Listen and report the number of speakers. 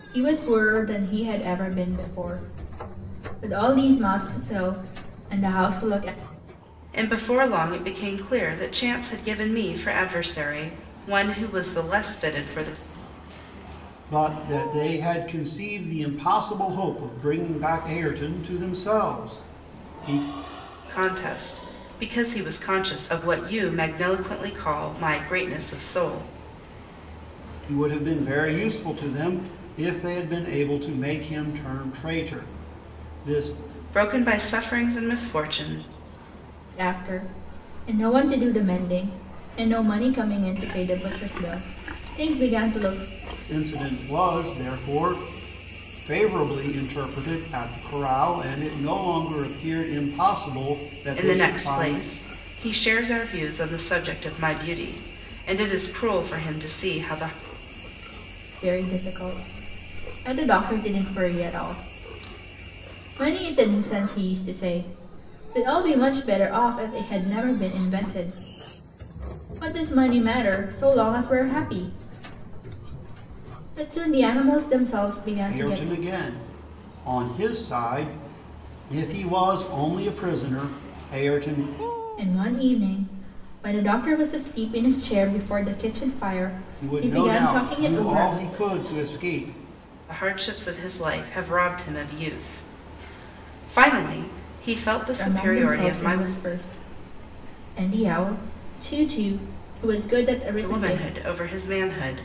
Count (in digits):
3